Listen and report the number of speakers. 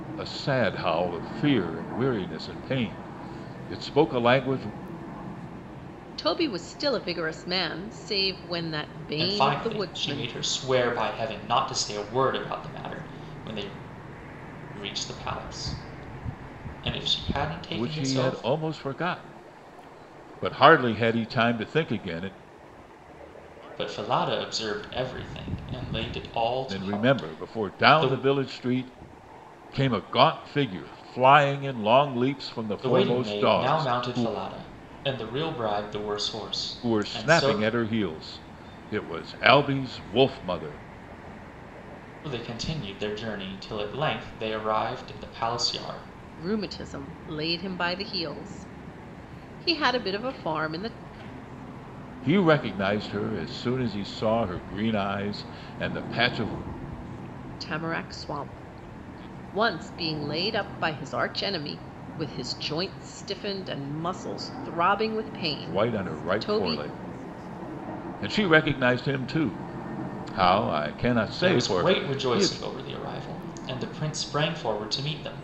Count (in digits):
3